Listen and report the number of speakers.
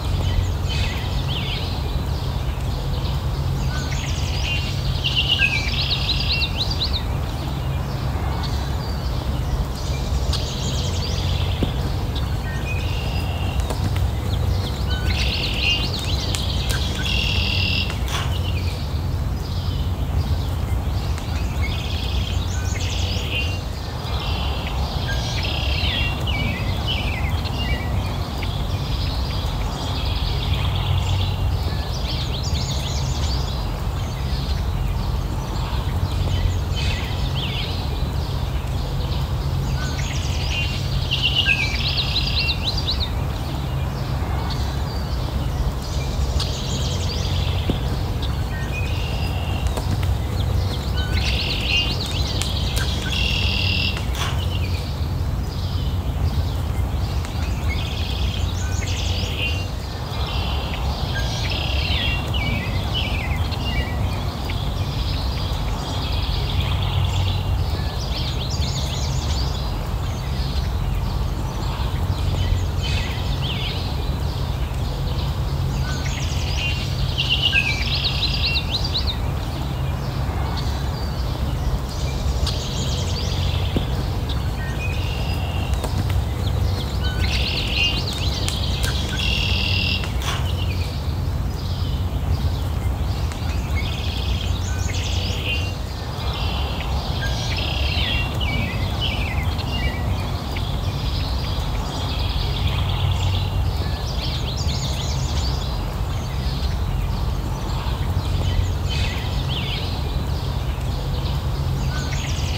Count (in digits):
0